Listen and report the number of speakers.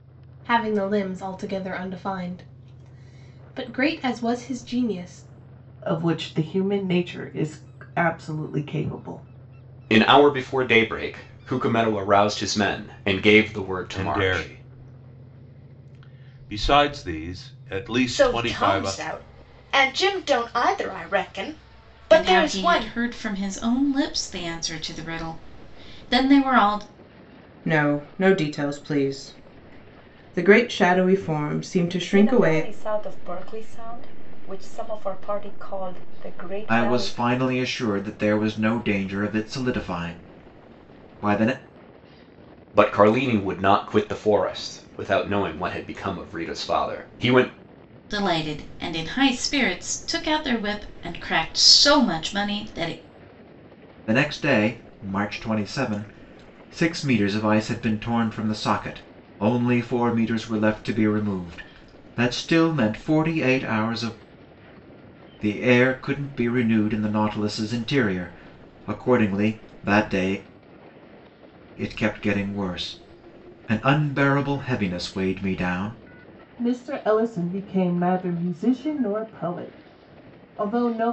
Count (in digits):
9